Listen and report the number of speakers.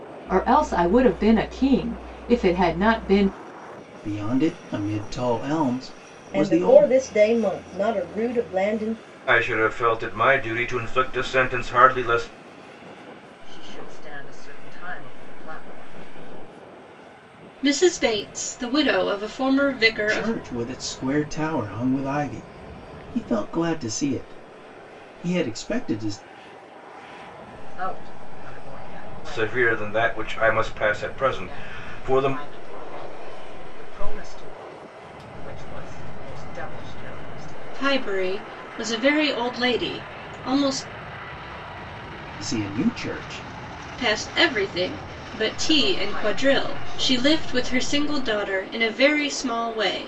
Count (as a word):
six